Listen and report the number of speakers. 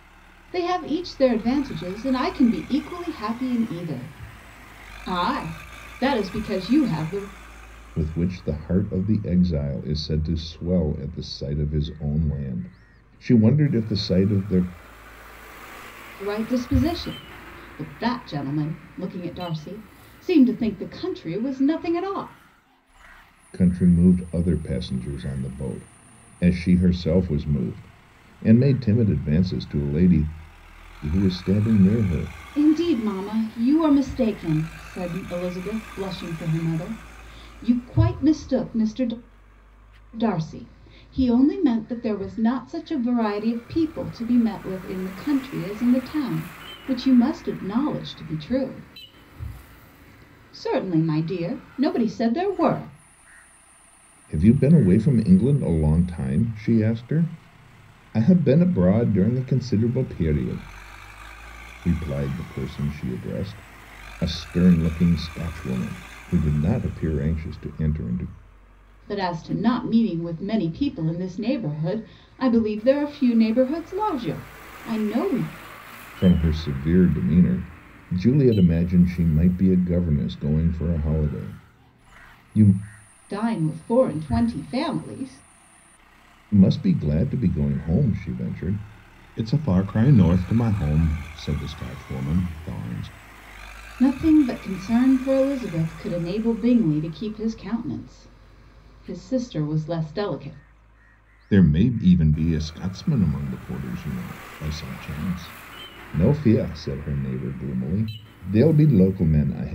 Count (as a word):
two